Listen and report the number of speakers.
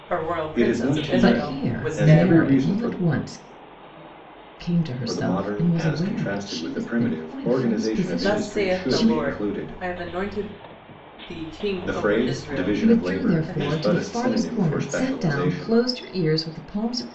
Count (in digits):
3